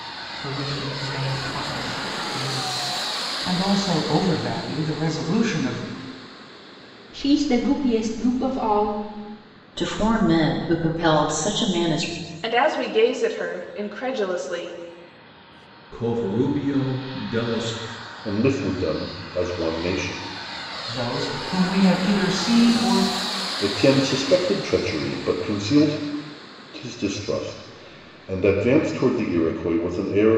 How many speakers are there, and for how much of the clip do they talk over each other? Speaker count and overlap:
7, no overlap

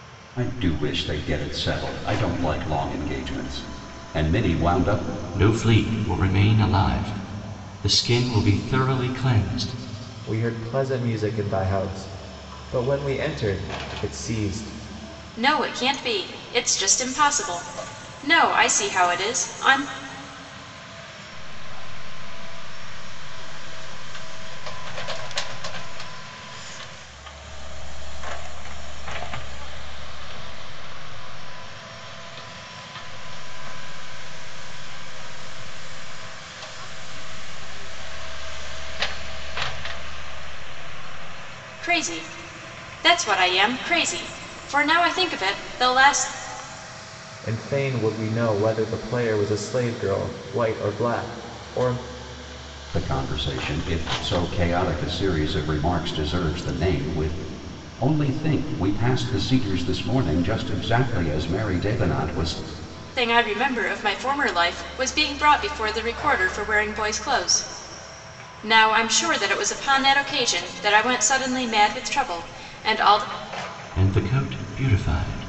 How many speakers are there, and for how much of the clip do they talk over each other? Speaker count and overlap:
5, no overlap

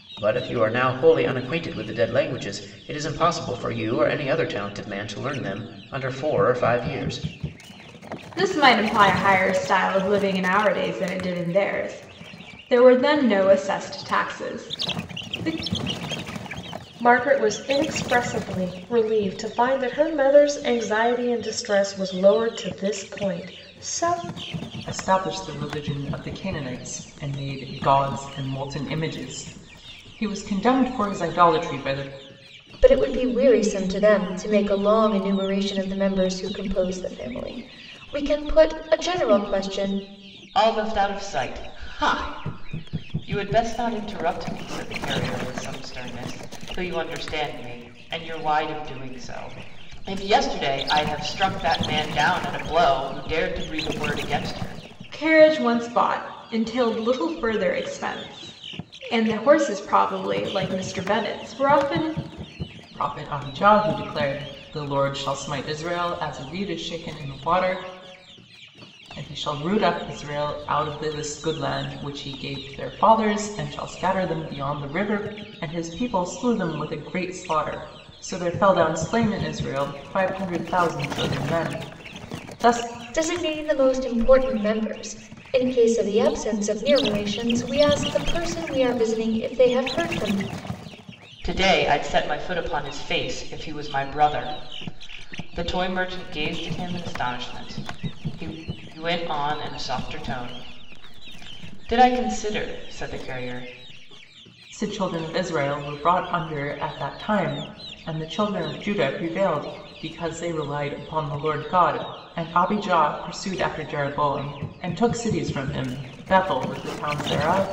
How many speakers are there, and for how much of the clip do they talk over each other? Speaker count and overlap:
6, no overlap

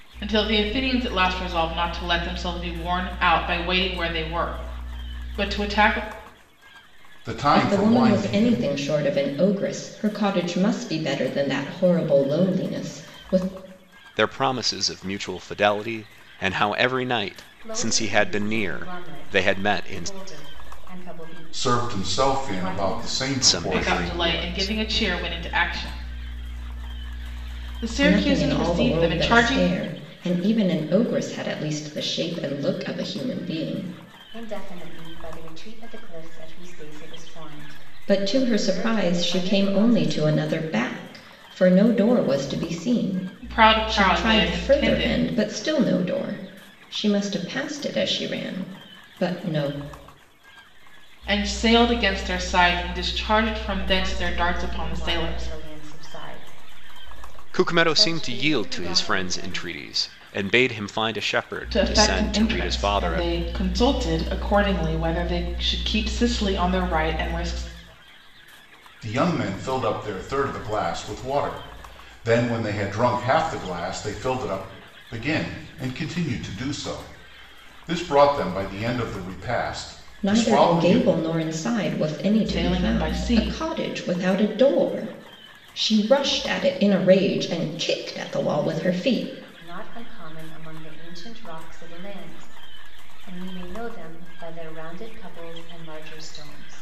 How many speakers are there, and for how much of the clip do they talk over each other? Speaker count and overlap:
5, about 21%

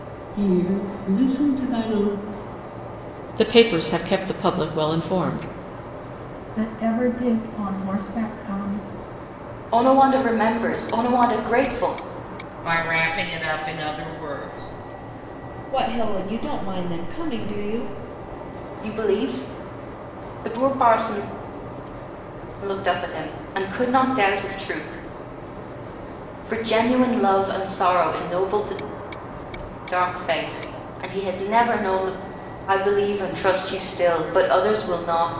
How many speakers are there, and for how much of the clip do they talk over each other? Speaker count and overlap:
6, no overlap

